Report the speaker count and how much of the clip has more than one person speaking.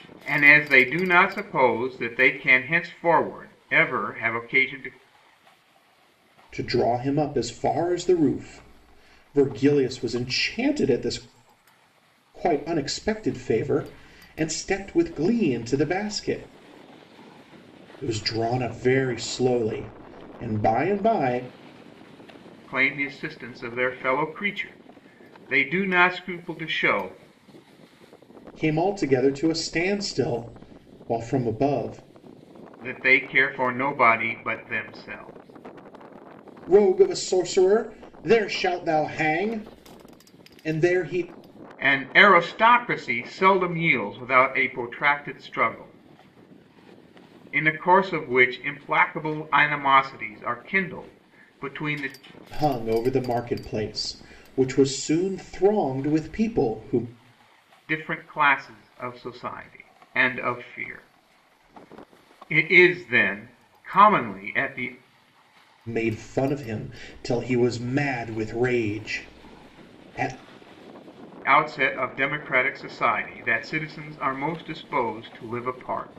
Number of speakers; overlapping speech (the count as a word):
two, no overlap